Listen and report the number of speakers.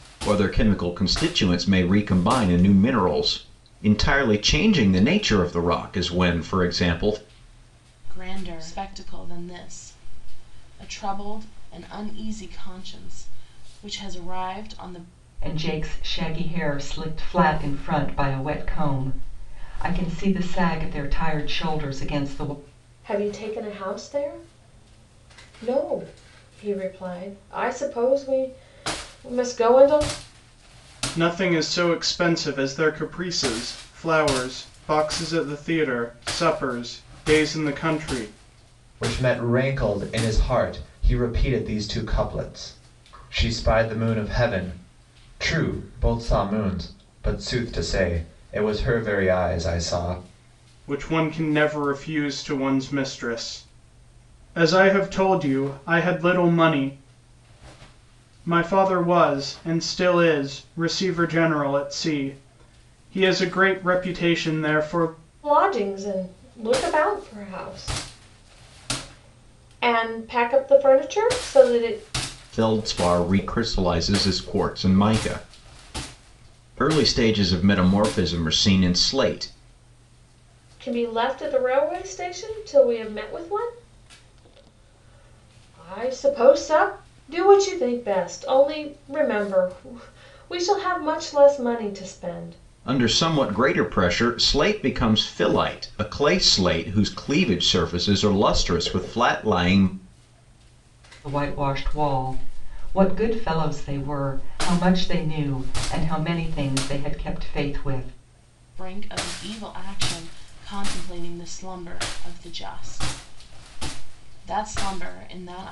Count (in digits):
6